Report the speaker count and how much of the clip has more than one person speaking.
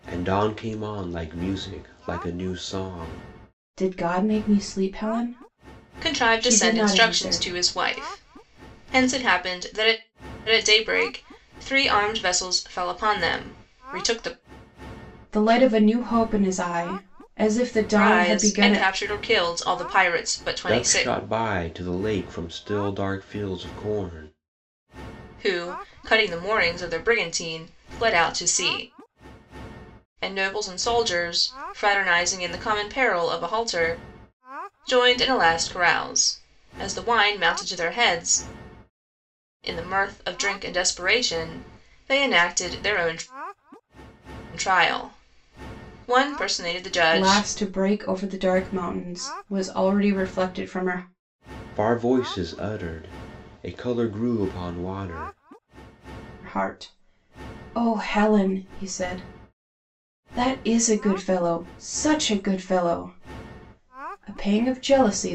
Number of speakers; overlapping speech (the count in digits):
3, about 5%